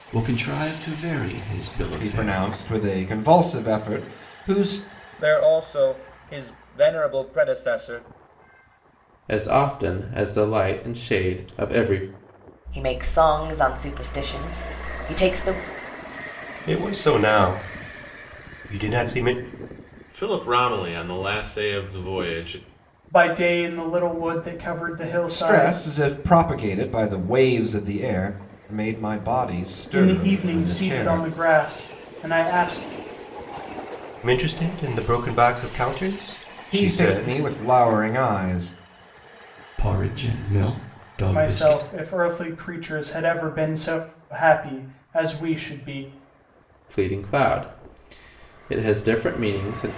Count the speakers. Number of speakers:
8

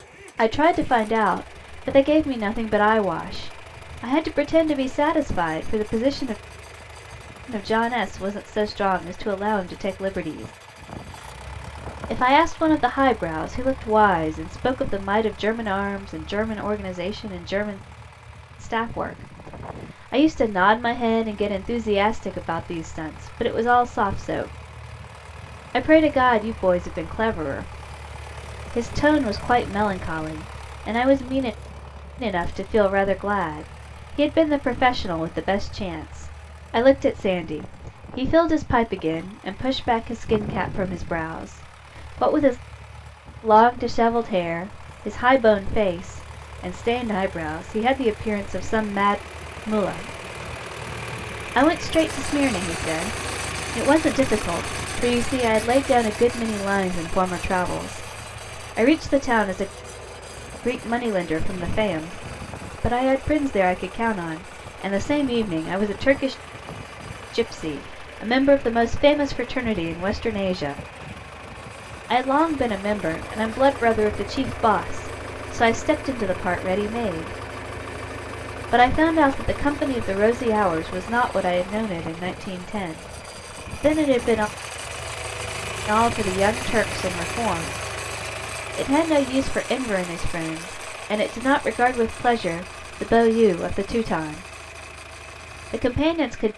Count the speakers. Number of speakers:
1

